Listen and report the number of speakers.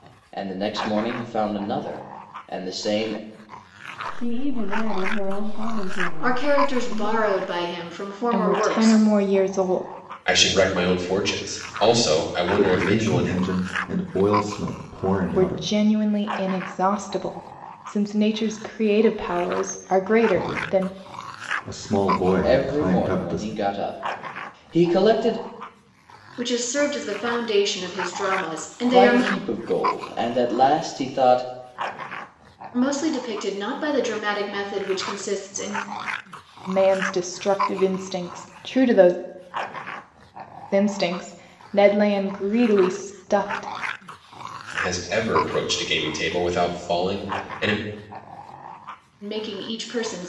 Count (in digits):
6